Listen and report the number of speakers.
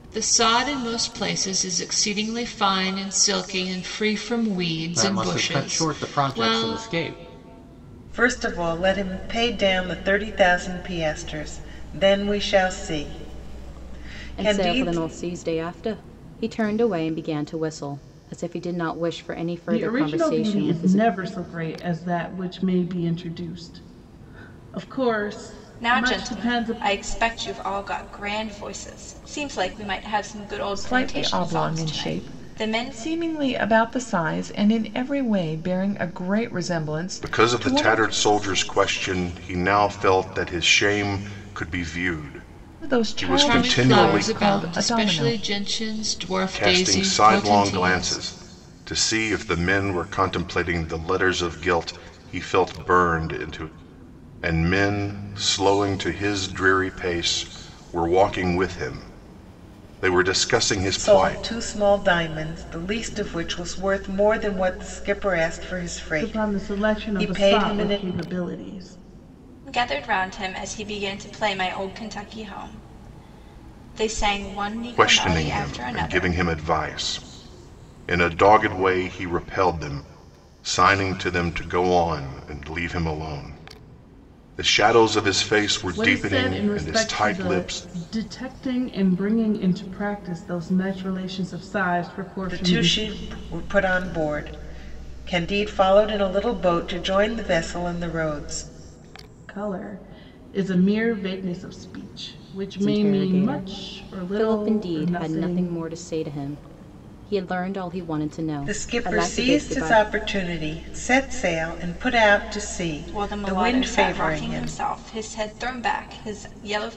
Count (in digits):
8